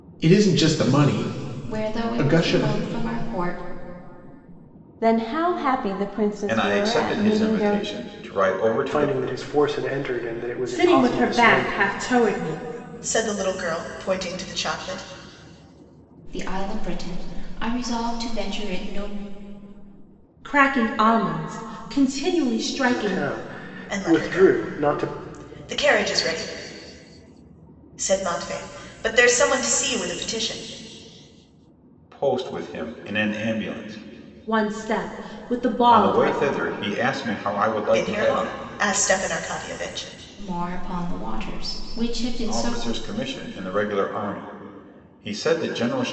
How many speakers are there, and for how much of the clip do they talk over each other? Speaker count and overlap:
seven, about 15%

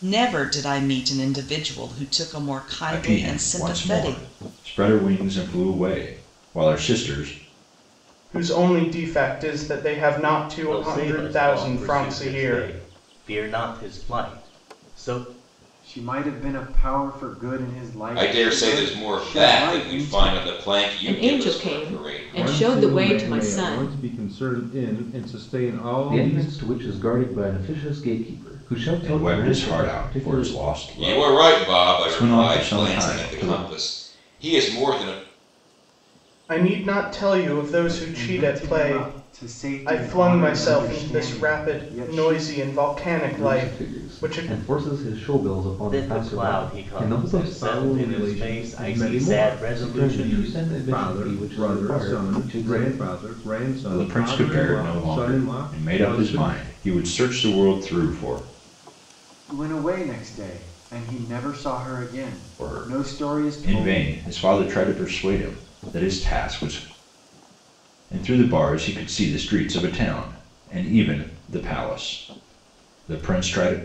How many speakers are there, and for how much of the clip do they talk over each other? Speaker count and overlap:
nine, about 40%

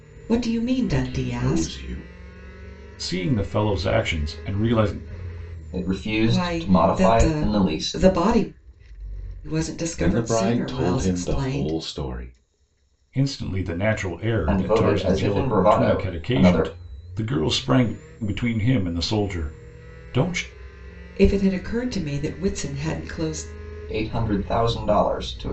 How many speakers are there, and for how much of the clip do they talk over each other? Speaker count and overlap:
four, about 27%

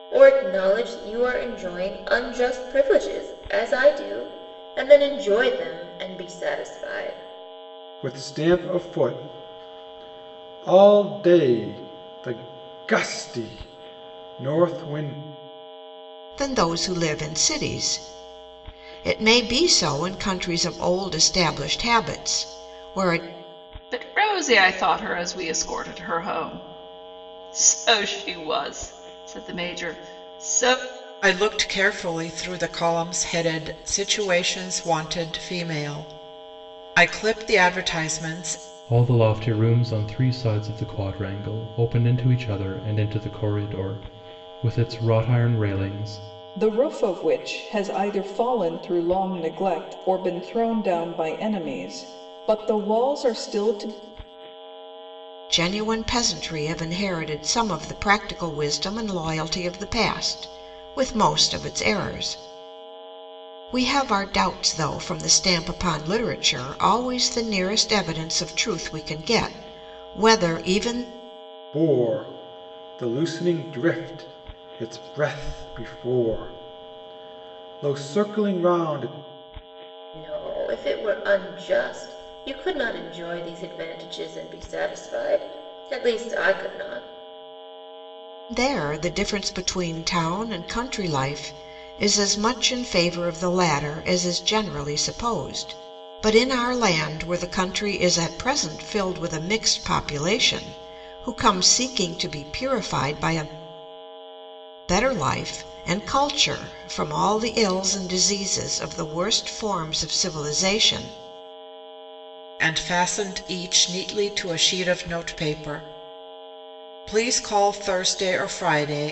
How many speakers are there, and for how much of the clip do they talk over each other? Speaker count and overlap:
seven, no overlap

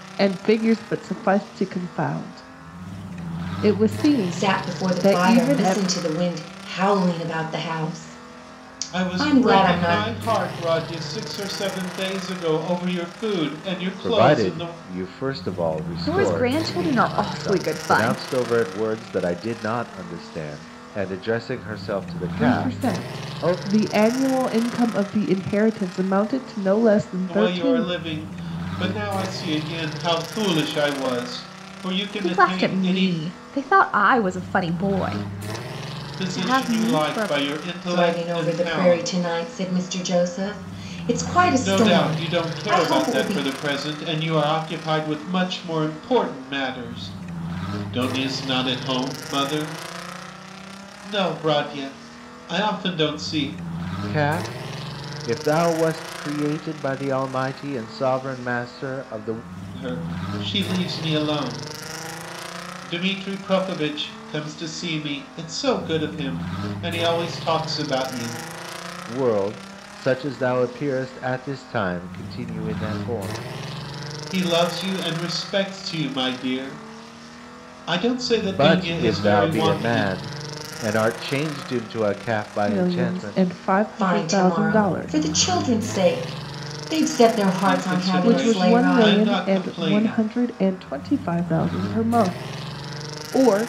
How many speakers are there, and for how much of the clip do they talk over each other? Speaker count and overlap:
five, about 21%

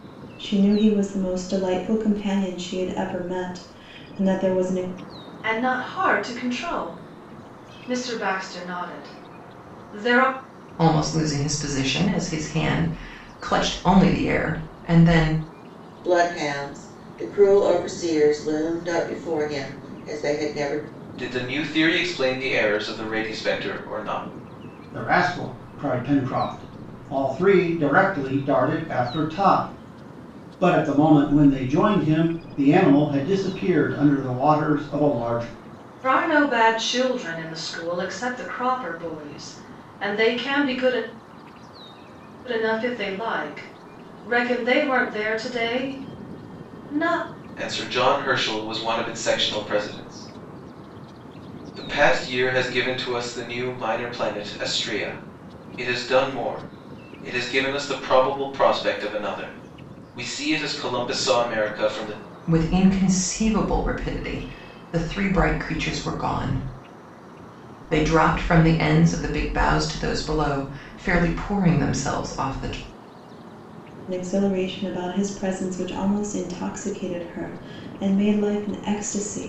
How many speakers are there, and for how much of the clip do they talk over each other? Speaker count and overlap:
six, no overlap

